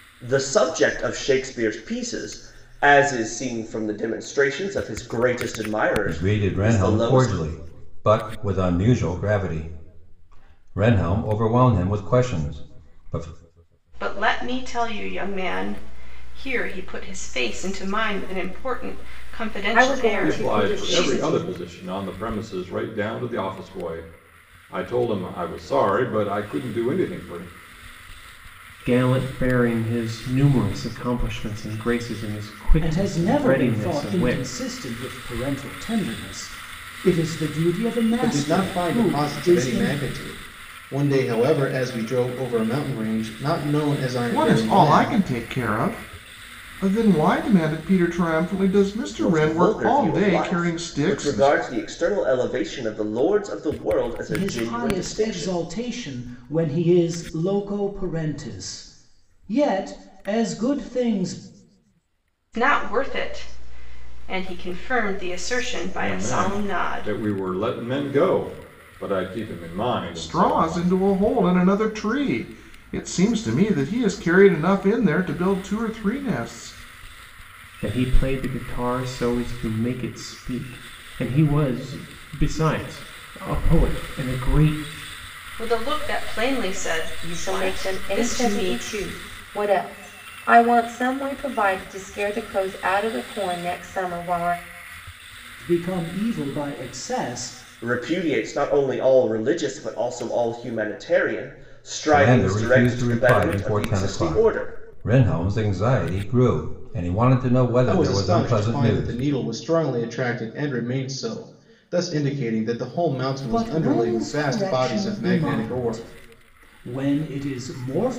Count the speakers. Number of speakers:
9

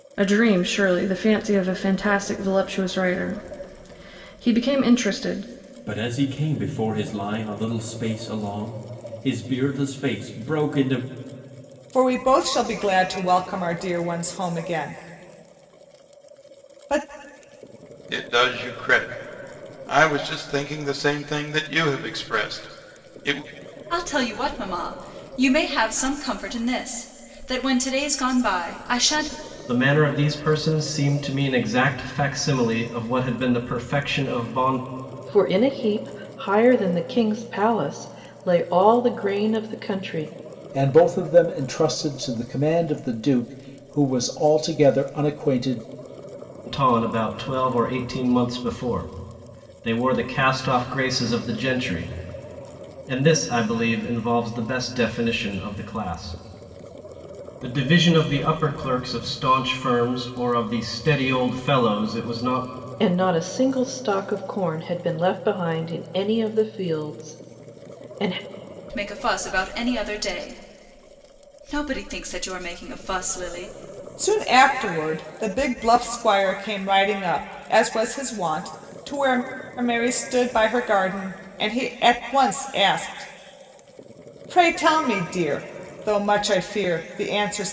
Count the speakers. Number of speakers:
8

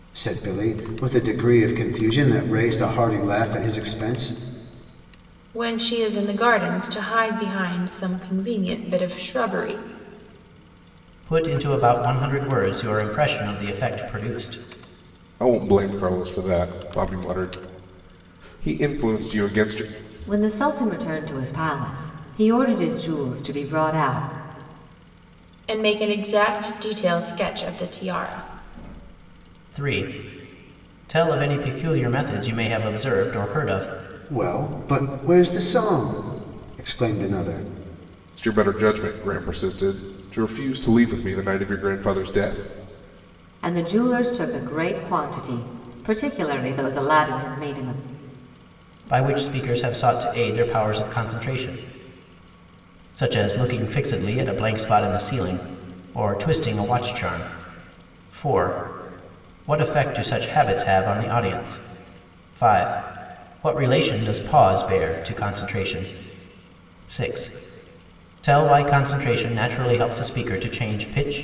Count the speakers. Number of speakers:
5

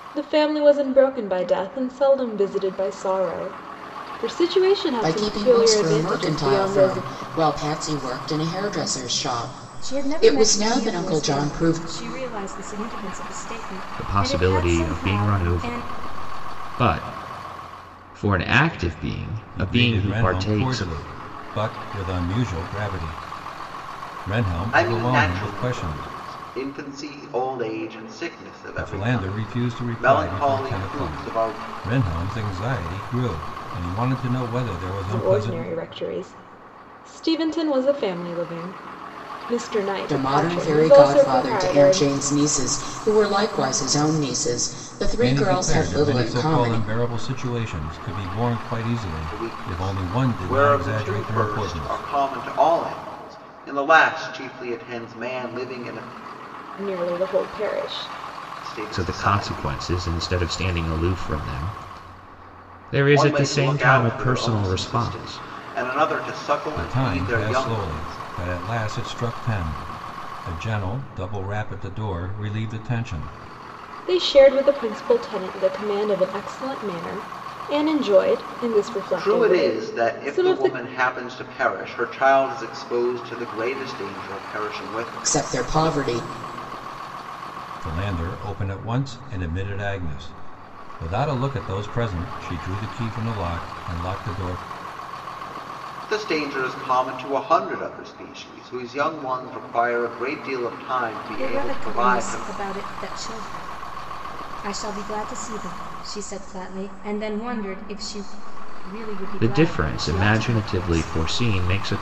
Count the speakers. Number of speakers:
6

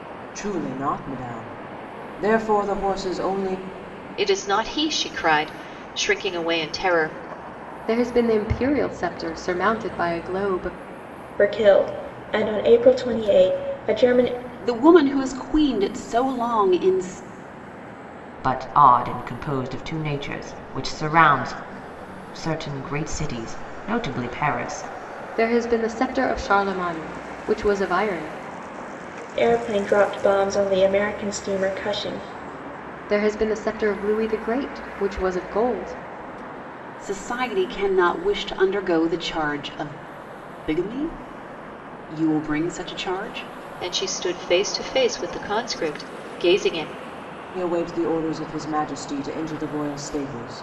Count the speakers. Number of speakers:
6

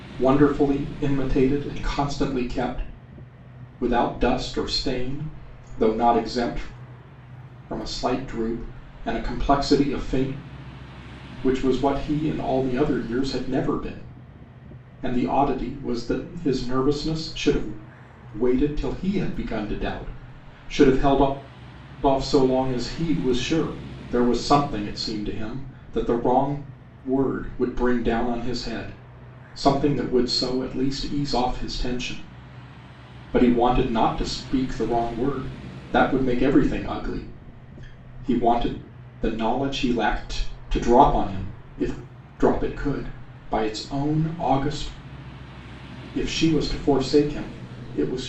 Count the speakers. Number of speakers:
1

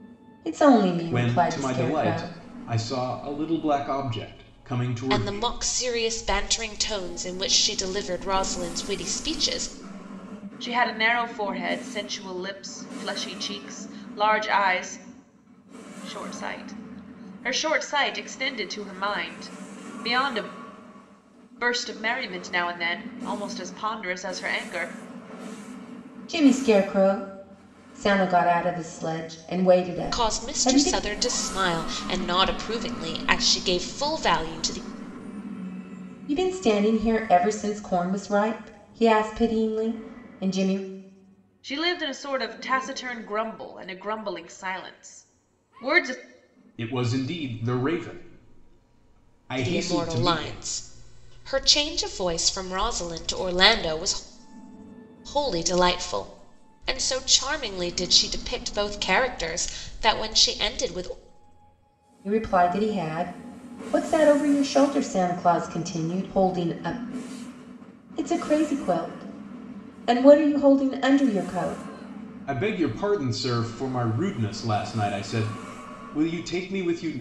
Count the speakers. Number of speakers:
4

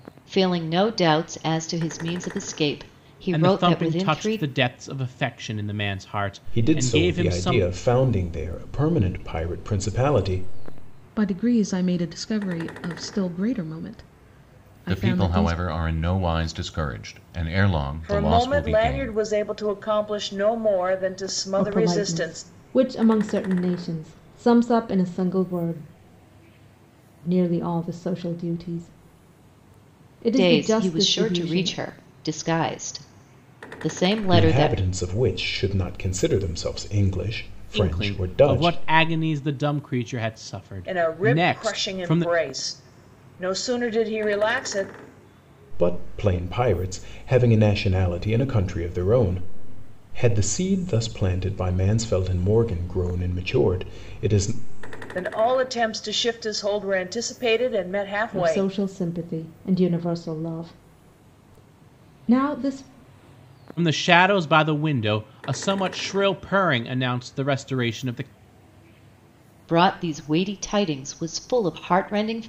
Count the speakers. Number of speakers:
7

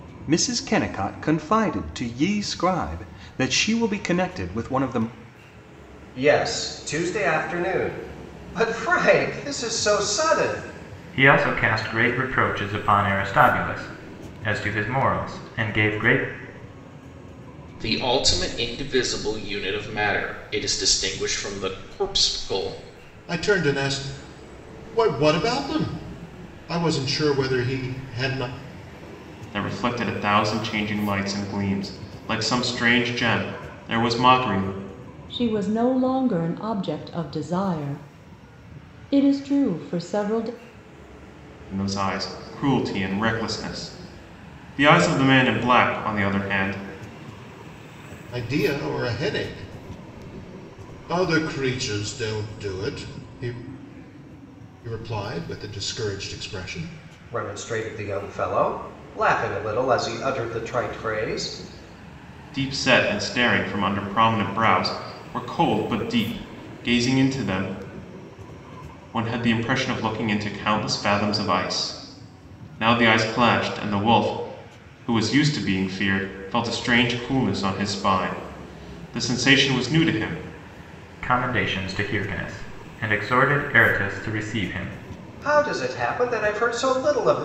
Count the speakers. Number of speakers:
7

